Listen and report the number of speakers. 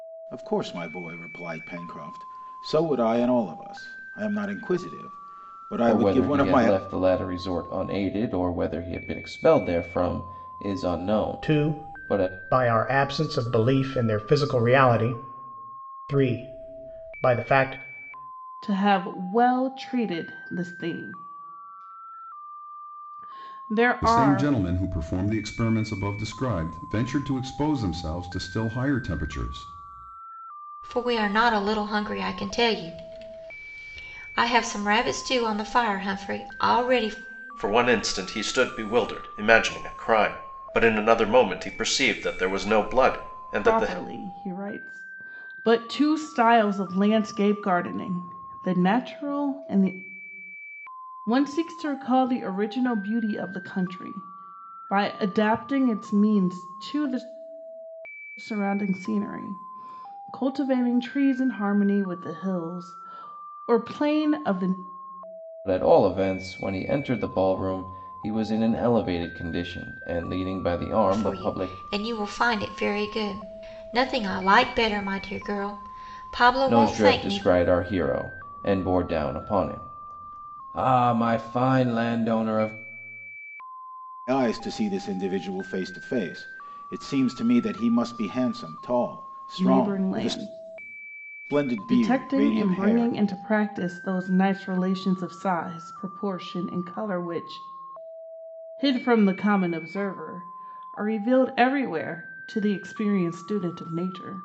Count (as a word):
seven